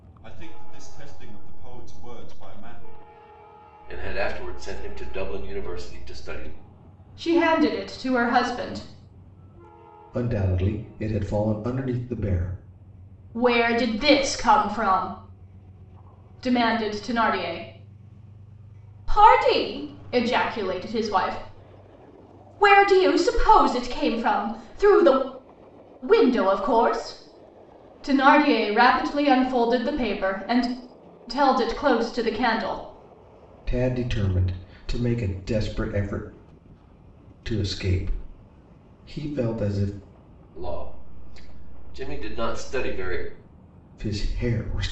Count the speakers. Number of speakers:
4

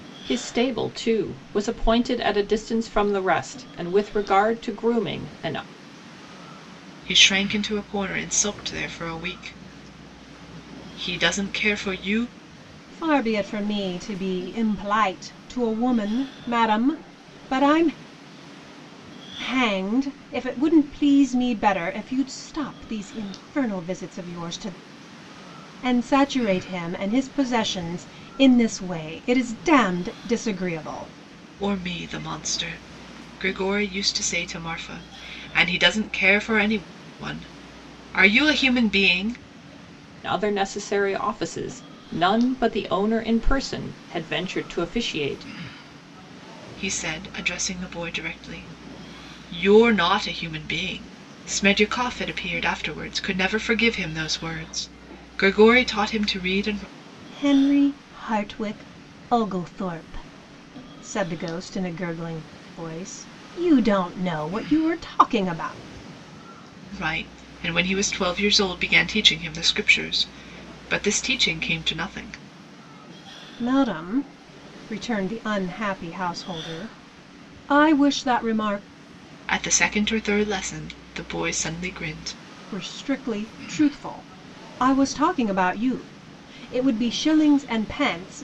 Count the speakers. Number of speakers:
3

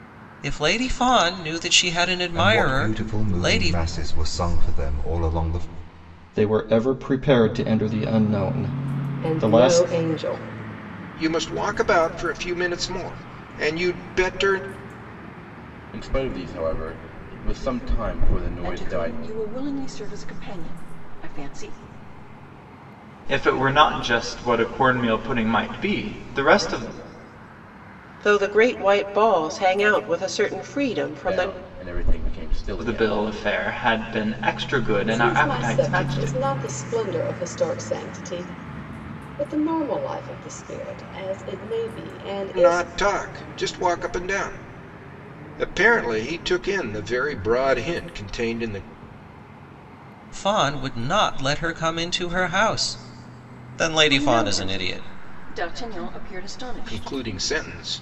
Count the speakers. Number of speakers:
9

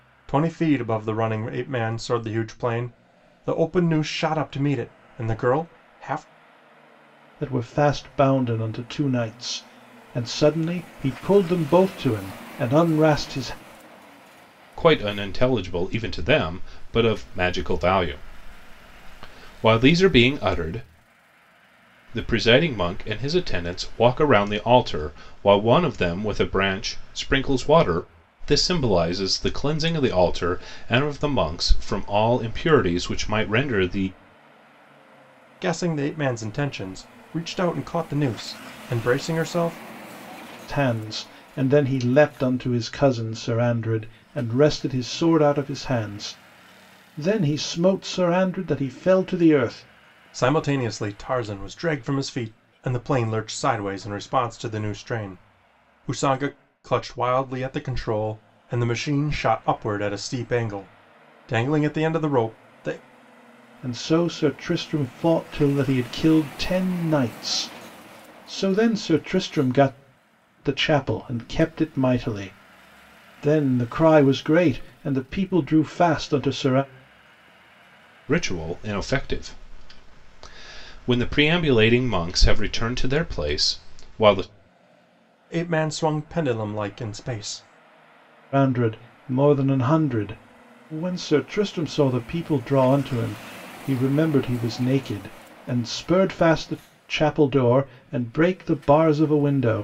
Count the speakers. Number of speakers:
3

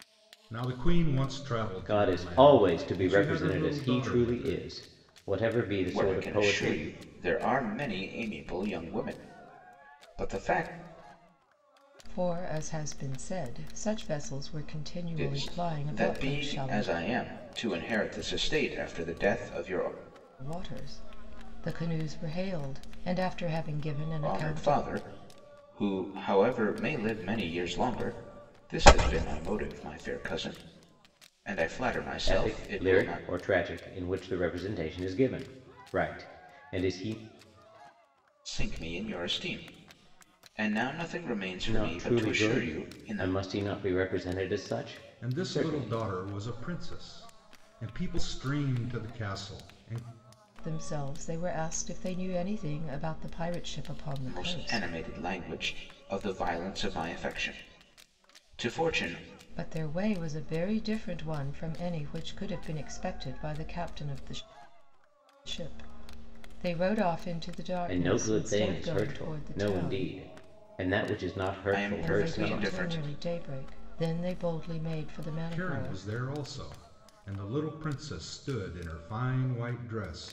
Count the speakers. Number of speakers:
4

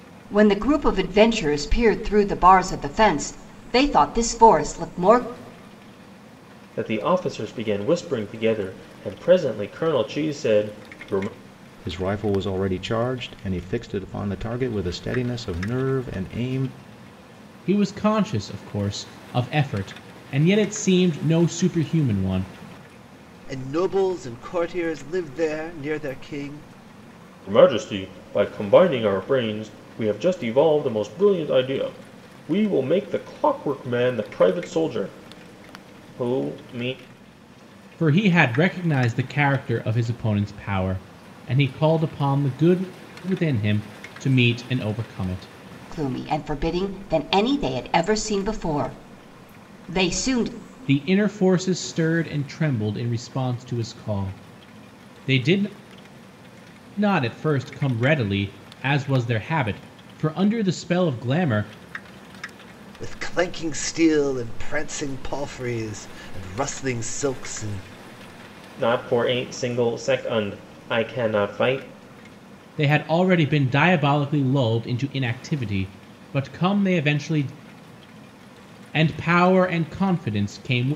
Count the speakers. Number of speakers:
5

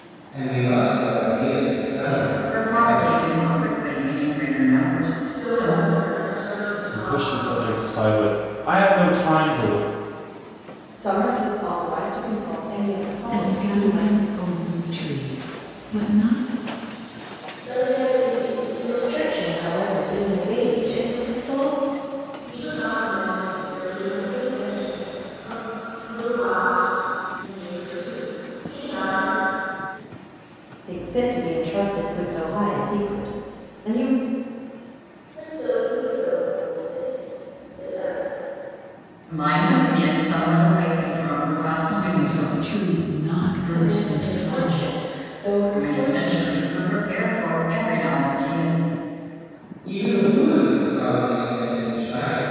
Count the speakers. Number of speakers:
8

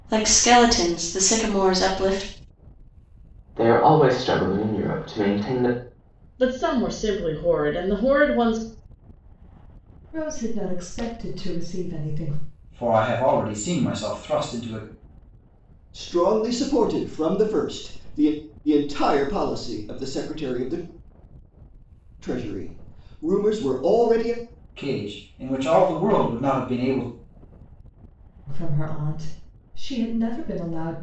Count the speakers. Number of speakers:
6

